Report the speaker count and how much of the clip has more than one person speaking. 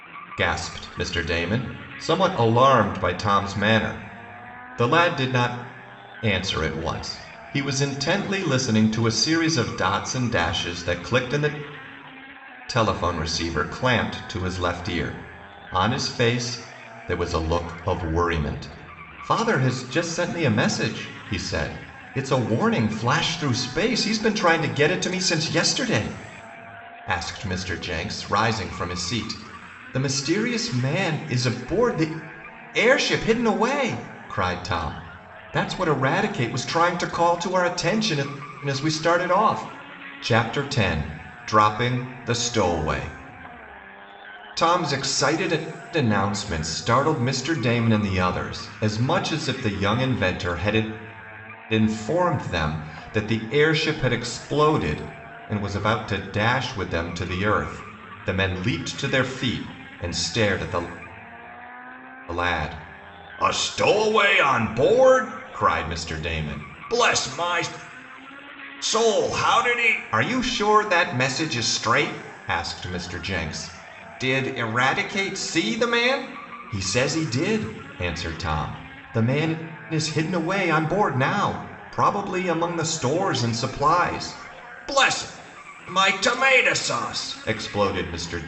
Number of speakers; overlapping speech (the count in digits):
1, no overlap